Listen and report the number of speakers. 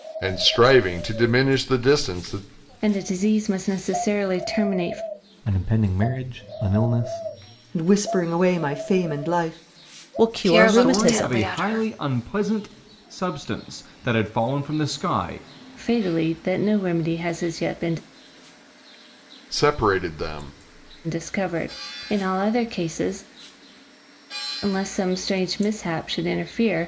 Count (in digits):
7